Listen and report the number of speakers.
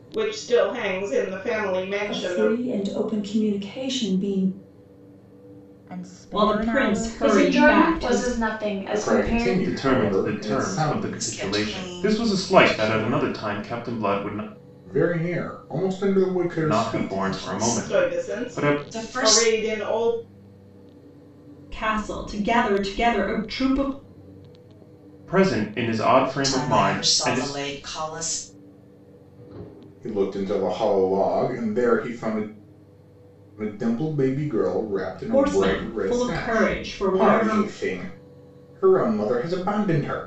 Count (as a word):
eight